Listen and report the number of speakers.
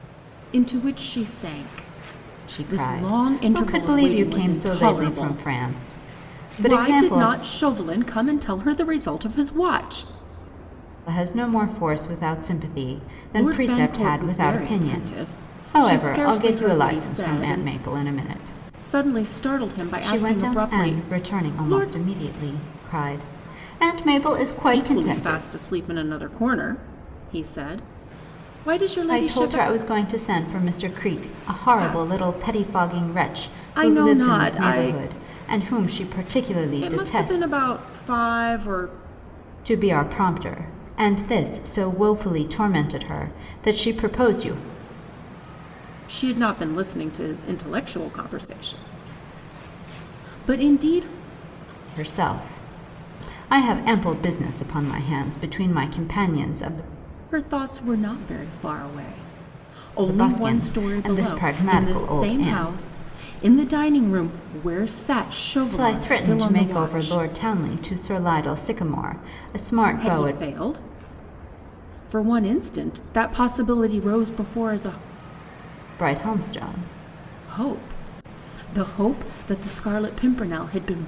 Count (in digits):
2